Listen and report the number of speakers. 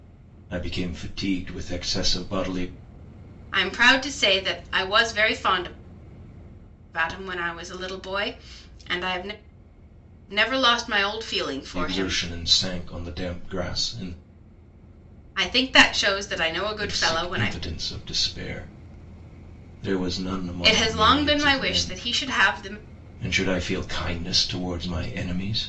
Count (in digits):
2